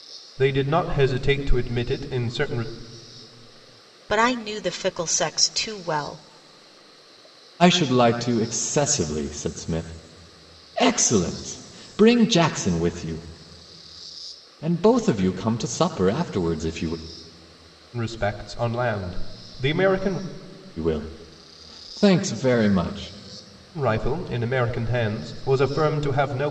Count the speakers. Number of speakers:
3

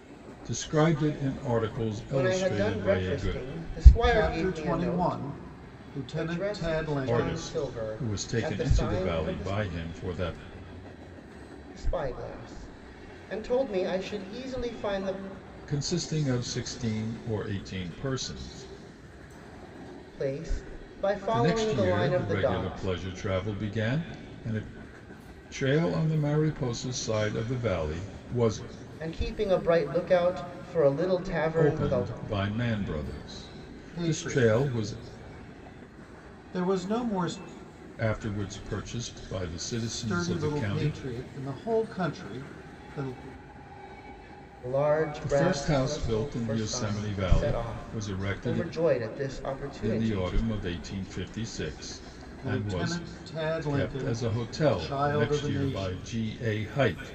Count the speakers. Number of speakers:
3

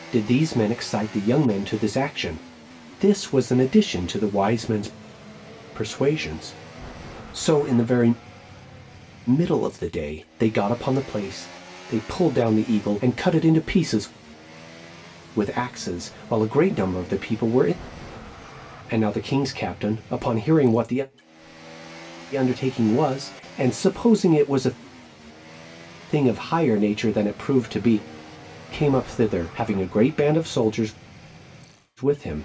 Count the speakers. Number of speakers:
1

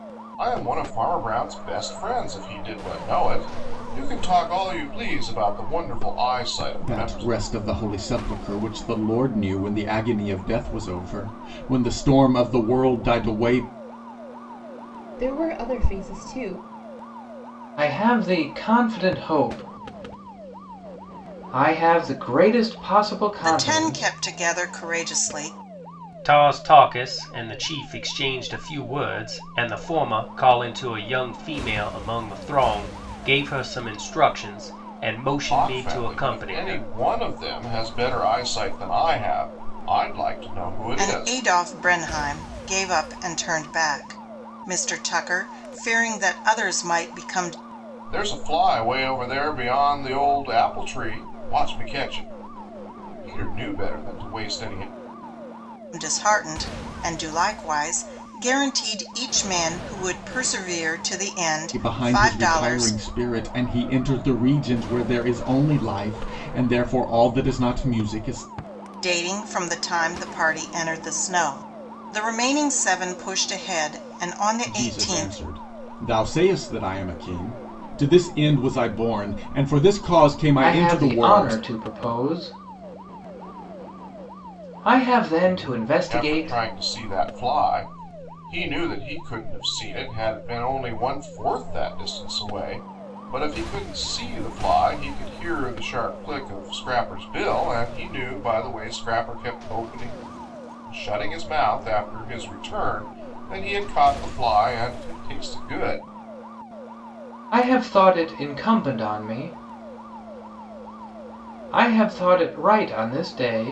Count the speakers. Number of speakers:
6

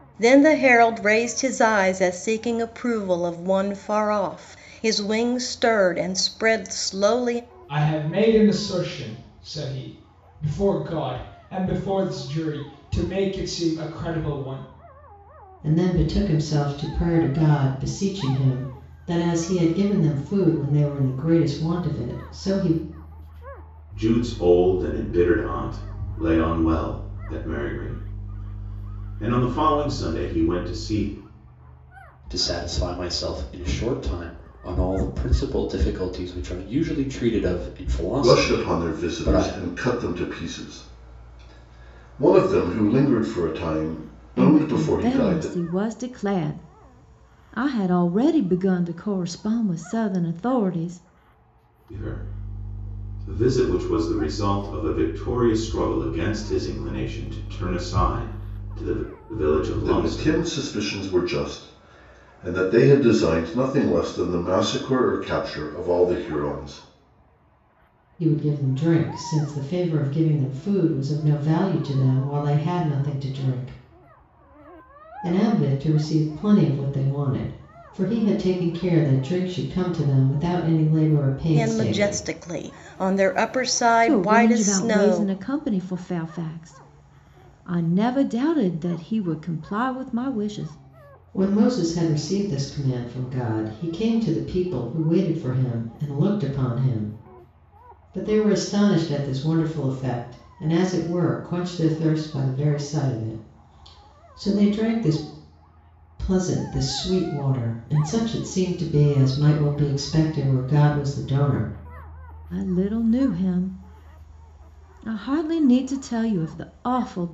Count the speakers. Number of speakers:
7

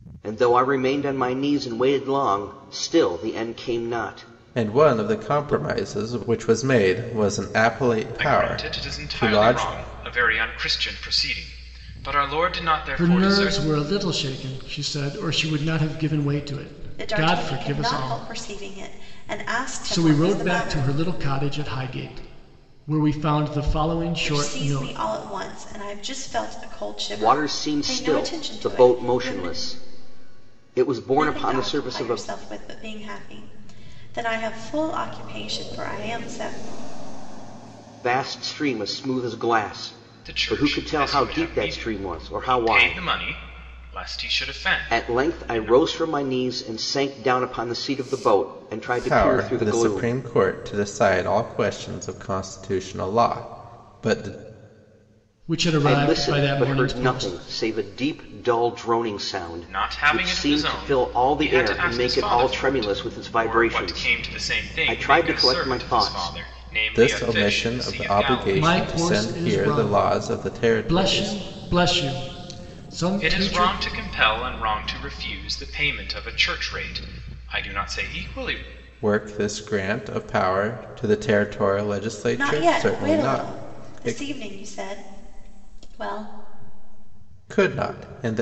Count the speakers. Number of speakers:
5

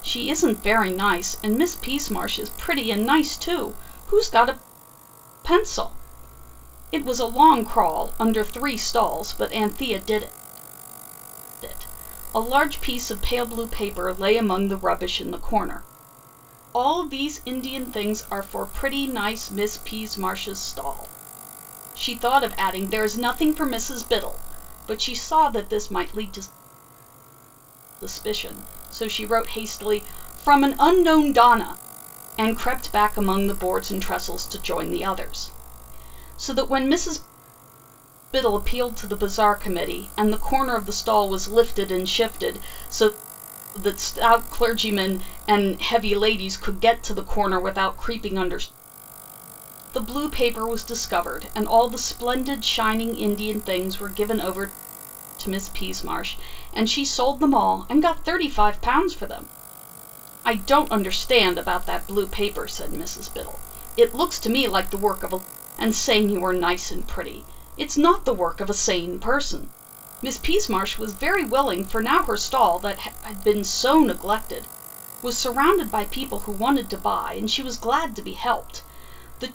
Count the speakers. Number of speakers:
1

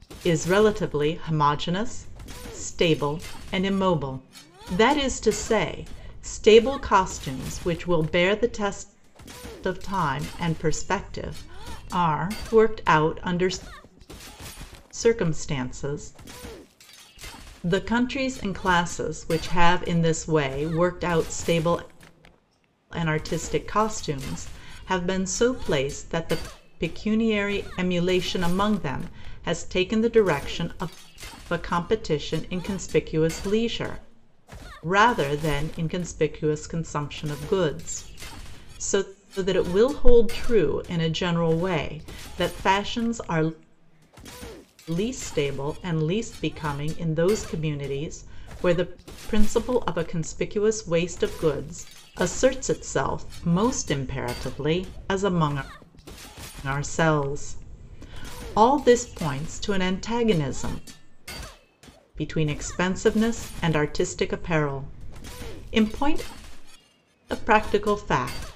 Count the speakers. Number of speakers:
1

